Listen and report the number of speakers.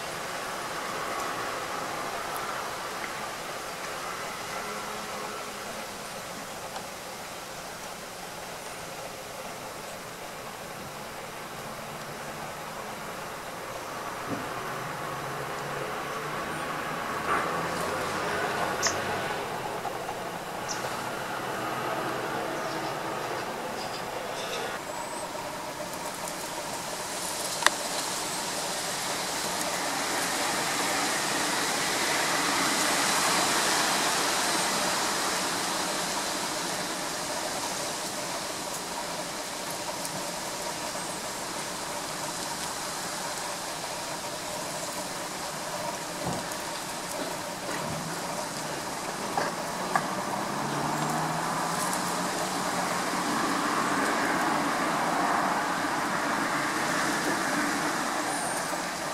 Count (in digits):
0